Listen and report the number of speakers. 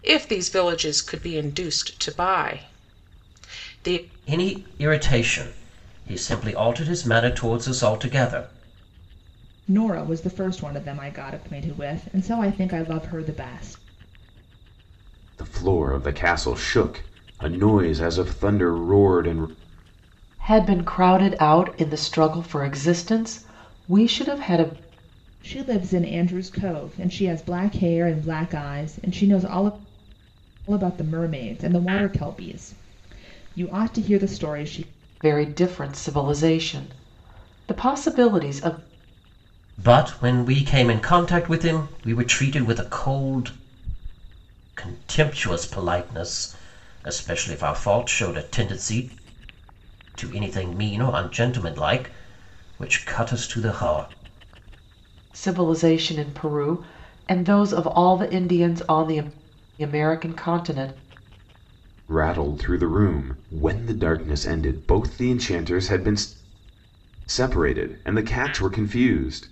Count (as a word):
five